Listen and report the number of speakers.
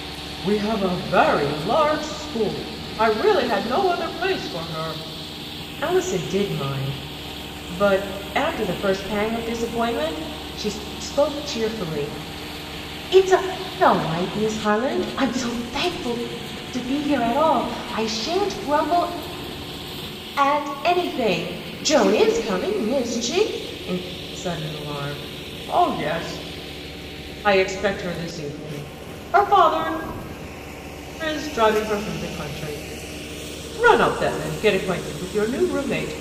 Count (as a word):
one